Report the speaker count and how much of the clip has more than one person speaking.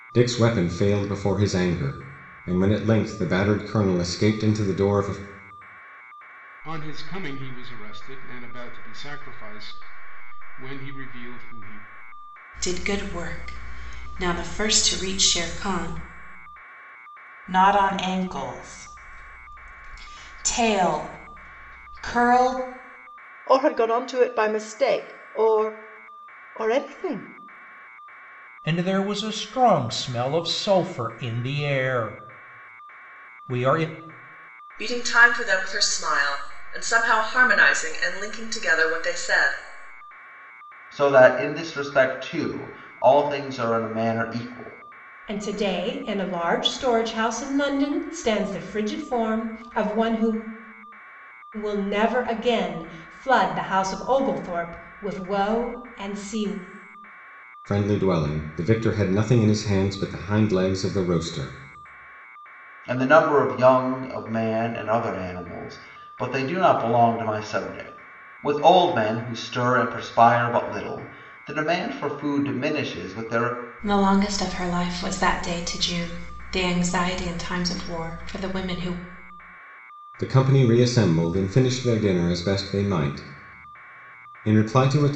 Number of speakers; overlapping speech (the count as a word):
nine, no overlap